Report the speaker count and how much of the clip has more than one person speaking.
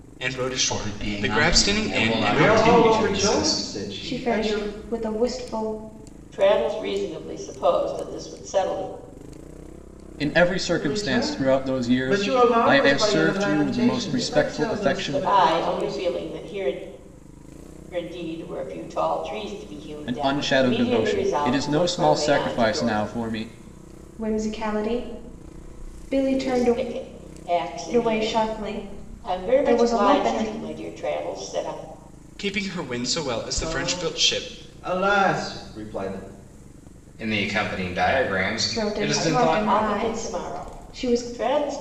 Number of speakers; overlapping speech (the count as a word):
seven, about 43%